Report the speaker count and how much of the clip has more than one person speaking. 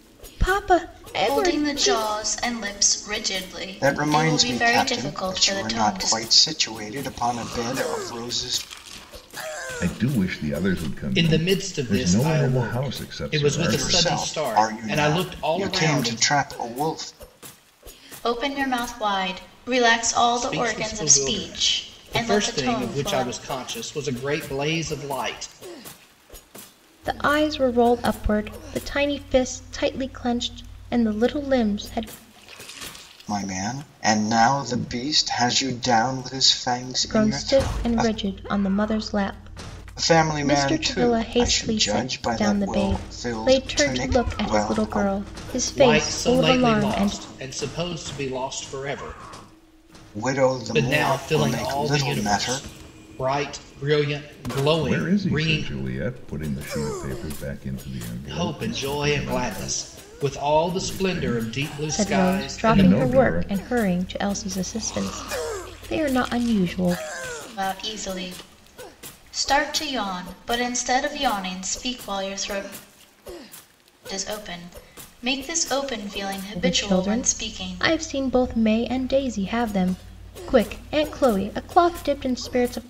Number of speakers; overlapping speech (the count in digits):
5, about 33%